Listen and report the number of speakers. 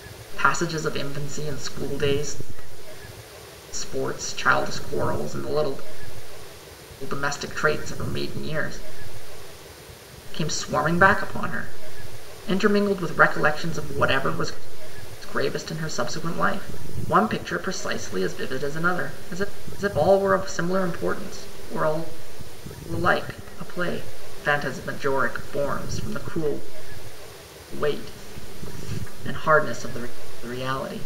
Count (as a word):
one